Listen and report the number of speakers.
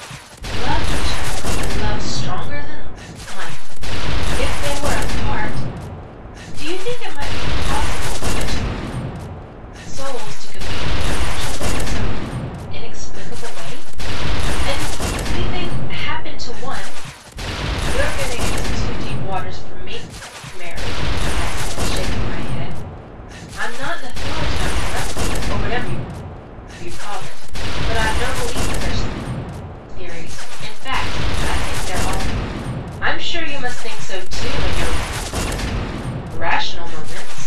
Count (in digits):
1